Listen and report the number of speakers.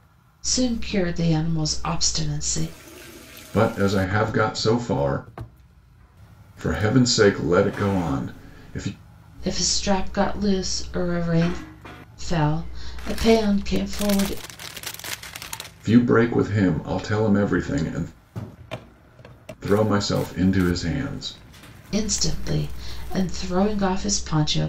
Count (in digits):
2